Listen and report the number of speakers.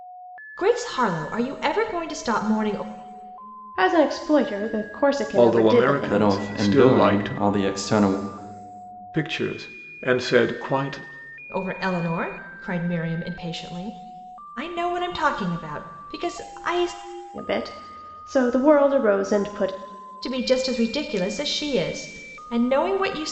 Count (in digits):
4